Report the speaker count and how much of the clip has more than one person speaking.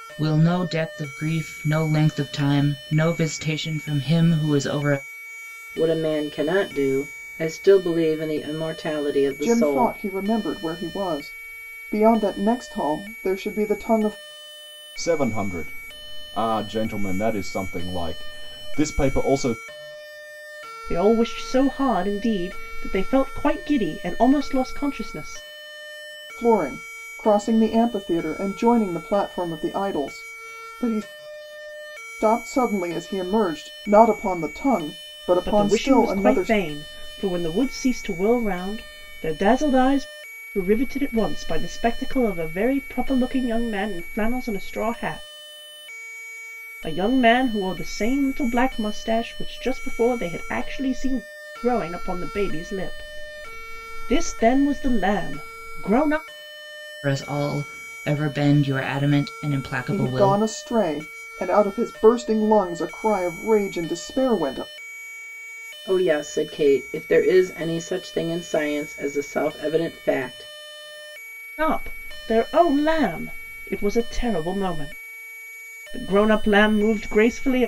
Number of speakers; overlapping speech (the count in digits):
5, about 3%